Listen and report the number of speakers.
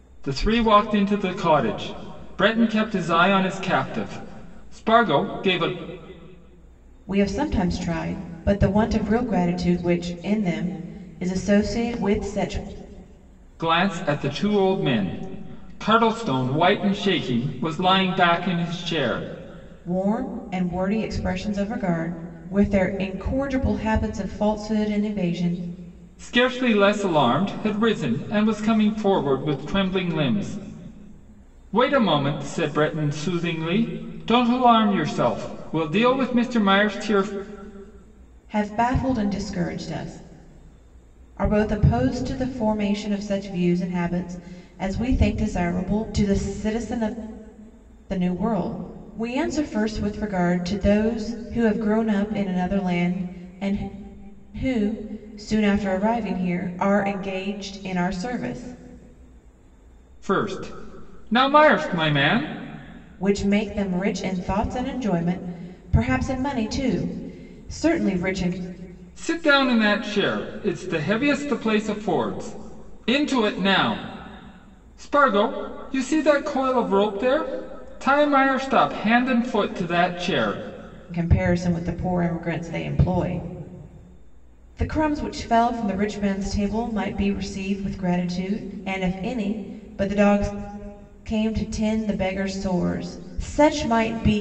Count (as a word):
two